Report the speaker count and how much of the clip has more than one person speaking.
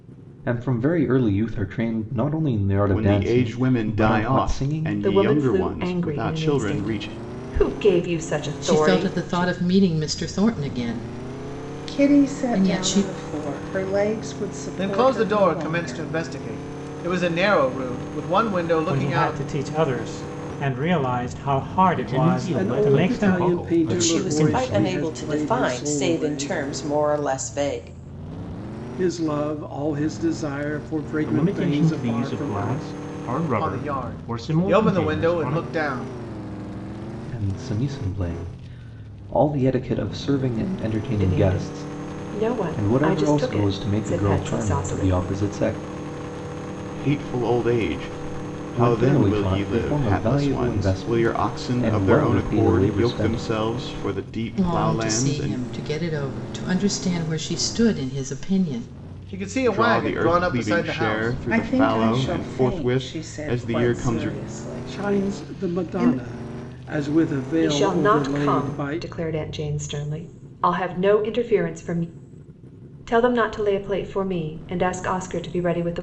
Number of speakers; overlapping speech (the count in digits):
10, about 44%